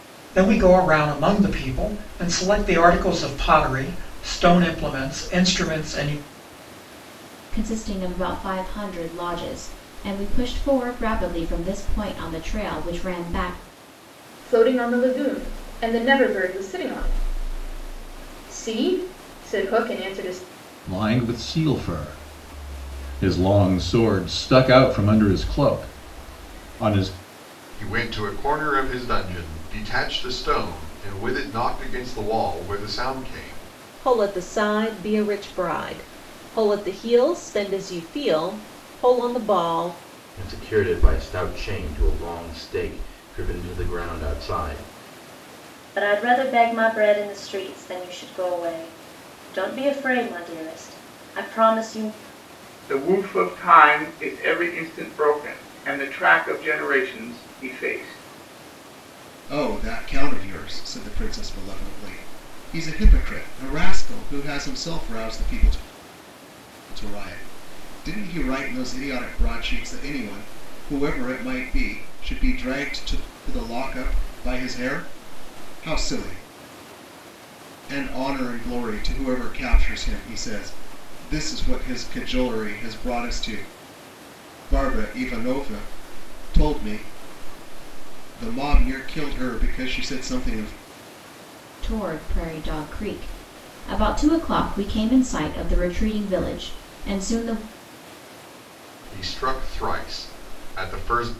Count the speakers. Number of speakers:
10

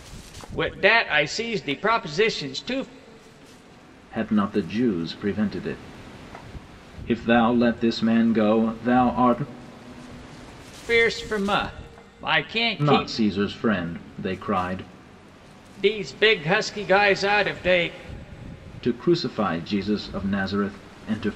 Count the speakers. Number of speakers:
2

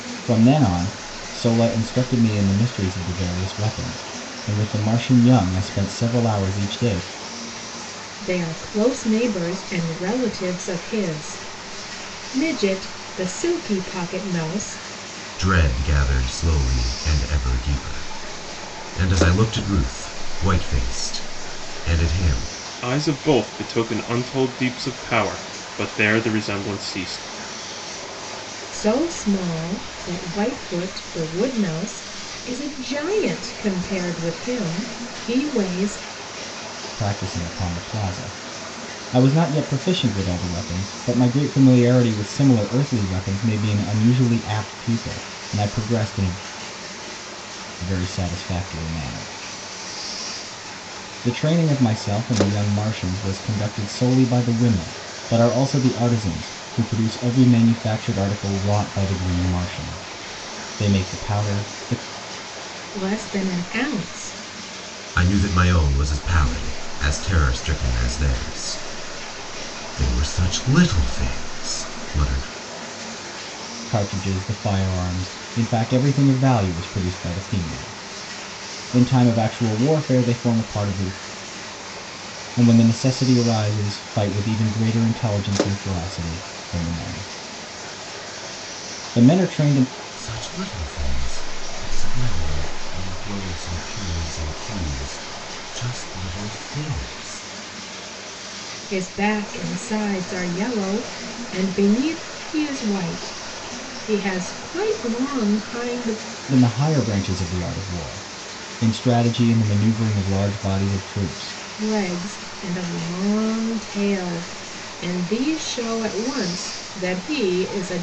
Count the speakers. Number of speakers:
4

